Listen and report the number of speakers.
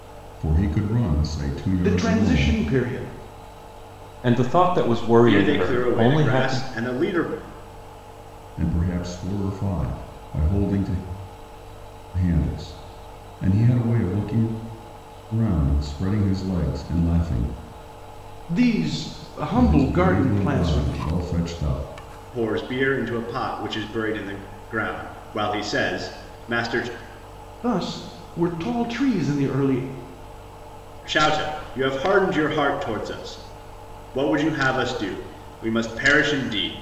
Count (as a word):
four